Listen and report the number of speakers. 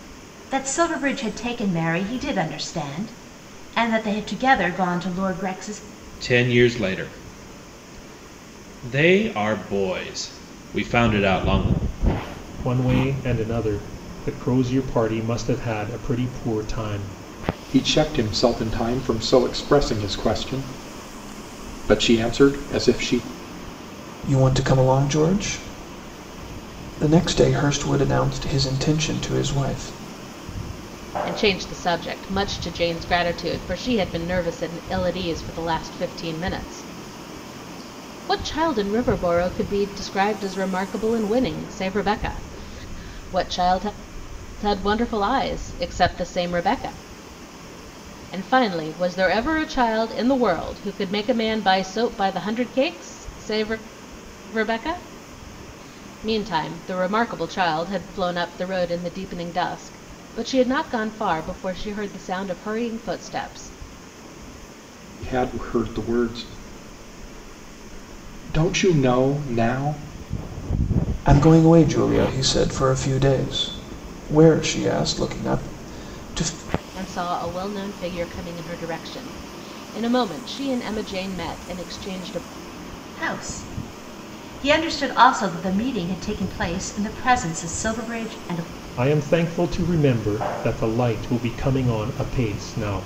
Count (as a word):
six